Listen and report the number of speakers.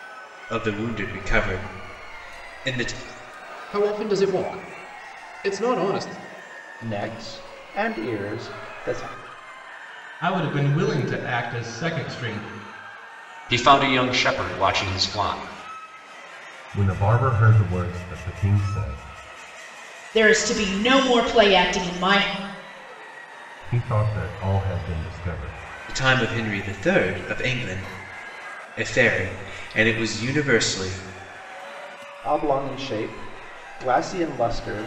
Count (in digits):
7